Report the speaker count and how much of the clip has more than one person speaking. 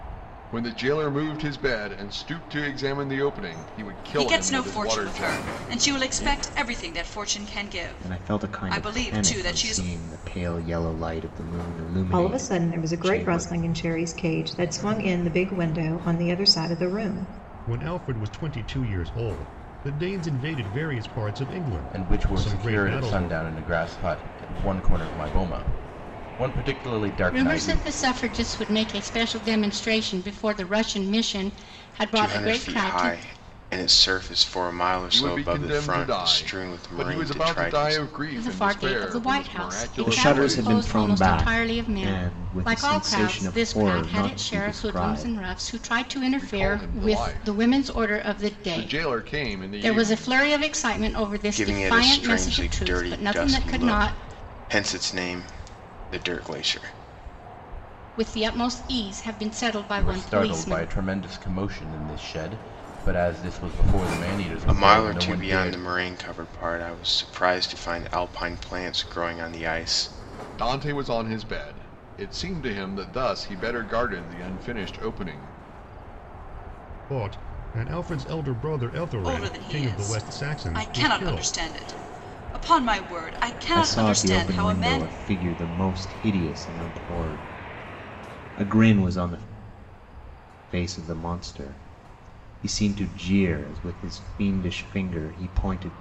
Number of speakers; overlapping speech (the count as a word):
eight, about 32%